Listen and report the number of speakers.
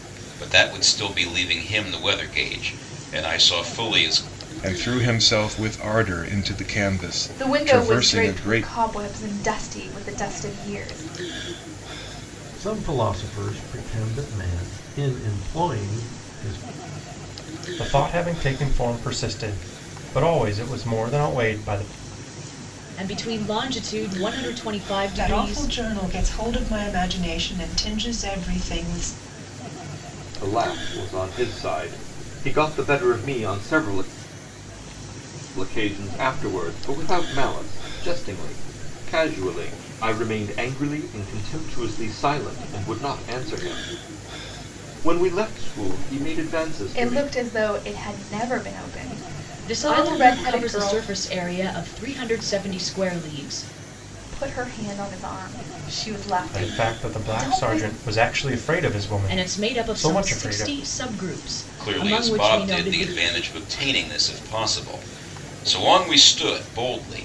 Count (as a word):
eight